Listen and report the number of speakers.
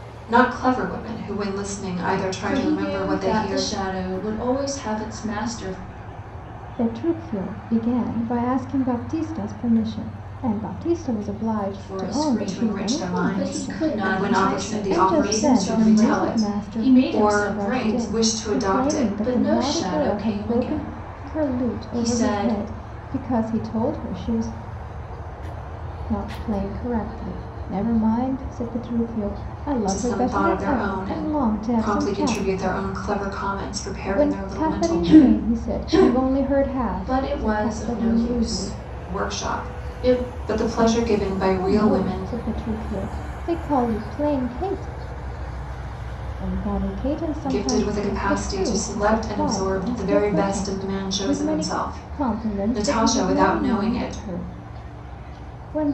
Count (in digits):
3